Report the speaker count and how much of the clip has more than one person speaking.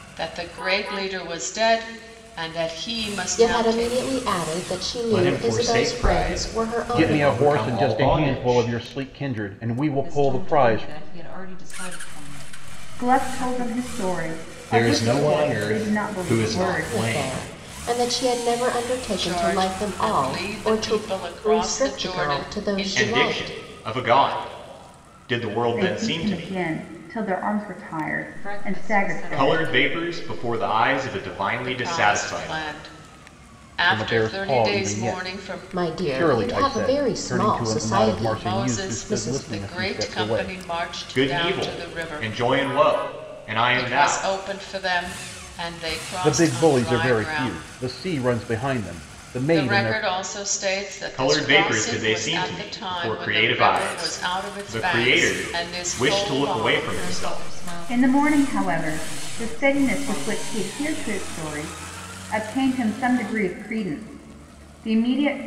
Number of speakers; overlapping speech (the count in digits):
6, about 55%